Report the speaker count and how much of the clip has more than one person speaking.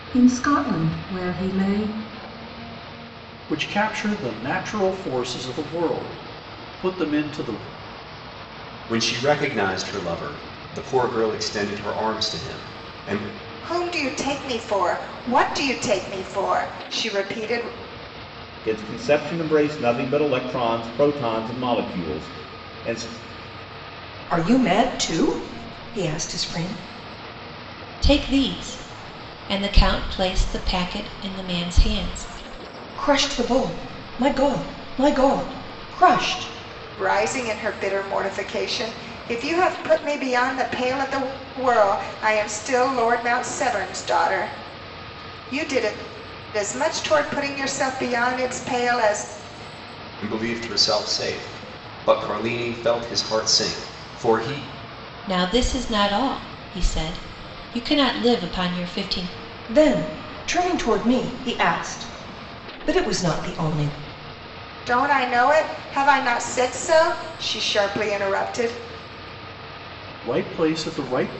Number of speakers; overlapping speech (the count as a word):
seven, no overlap